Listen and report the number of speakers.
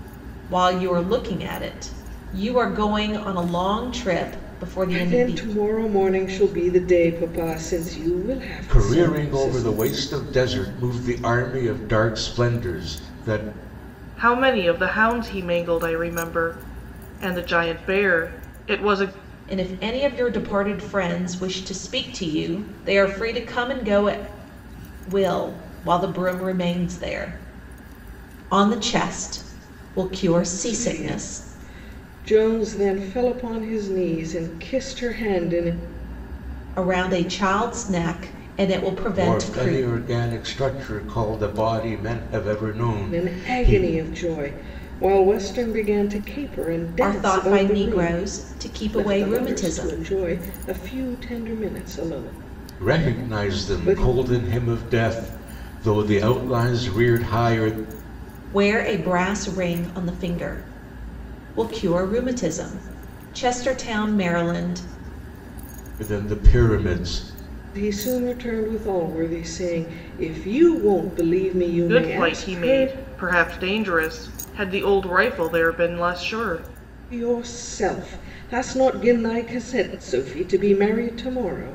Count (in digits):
4